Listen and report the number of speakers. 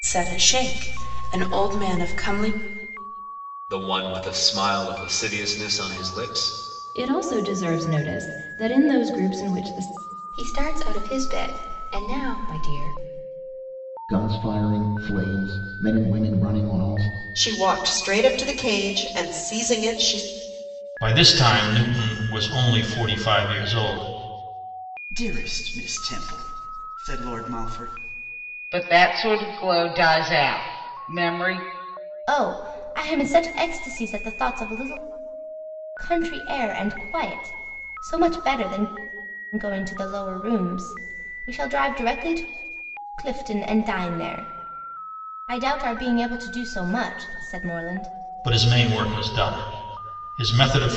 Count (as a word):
ten